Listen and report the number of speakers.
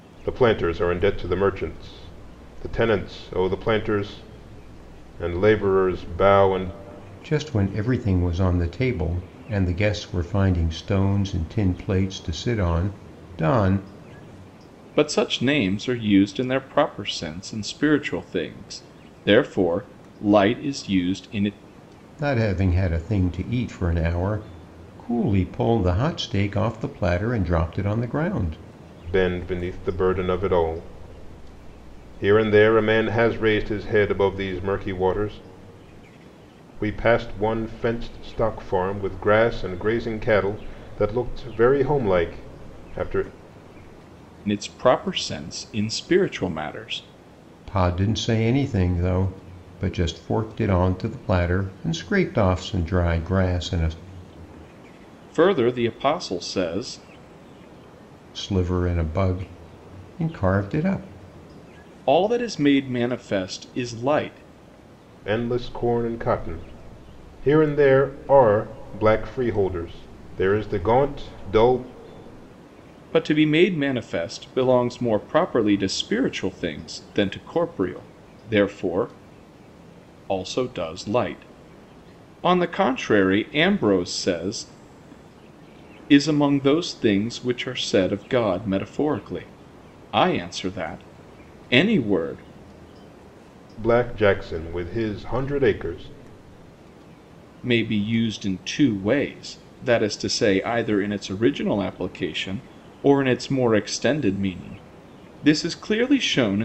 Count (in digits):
3